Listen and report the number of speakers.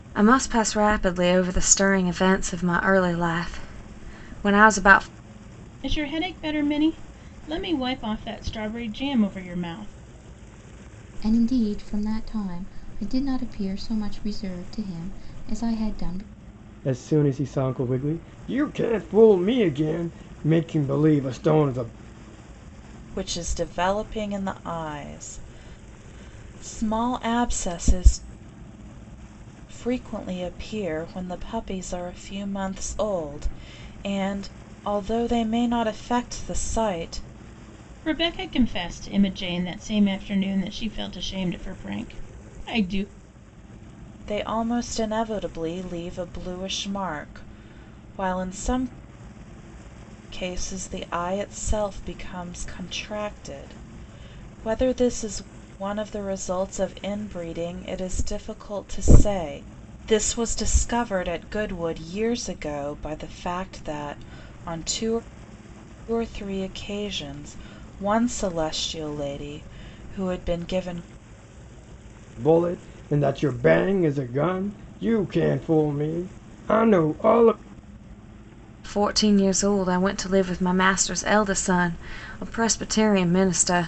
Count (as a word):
five